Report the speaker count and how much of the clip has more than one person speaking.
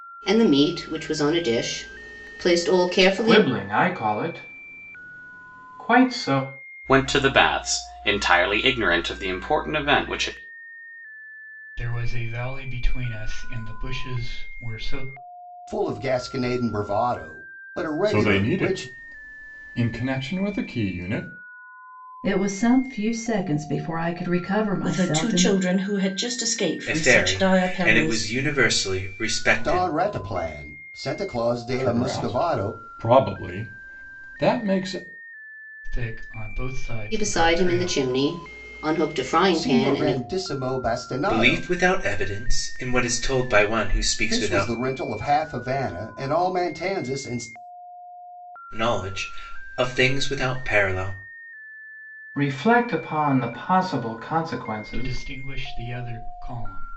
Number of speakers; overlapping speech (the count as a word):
nine, about 14%